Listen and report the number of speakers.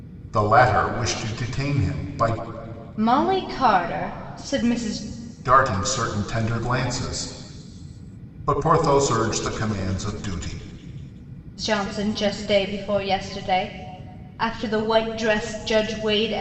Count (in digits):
2